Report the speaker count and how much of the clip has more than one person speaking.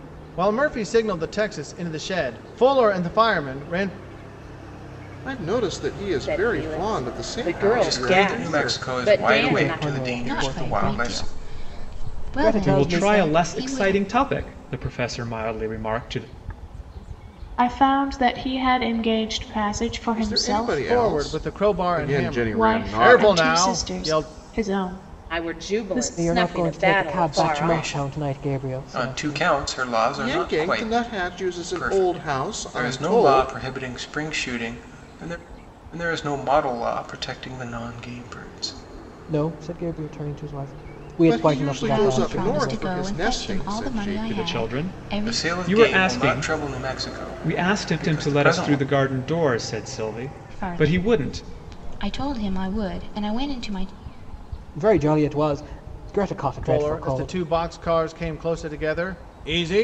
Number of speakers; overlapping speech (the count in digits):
8, about 47%